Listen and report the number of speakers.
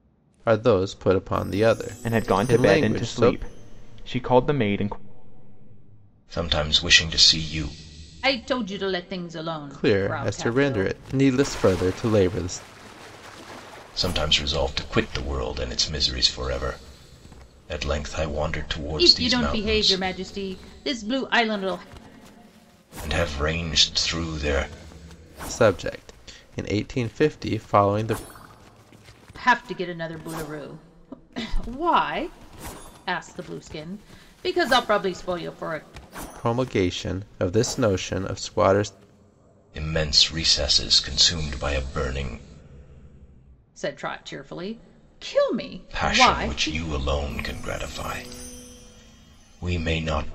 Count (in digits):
4